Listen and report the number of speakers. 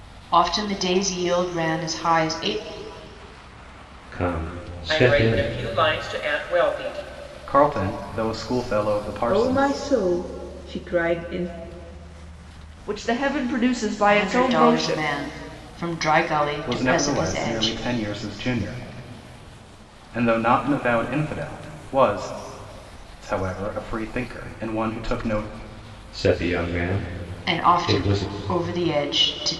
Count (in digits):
6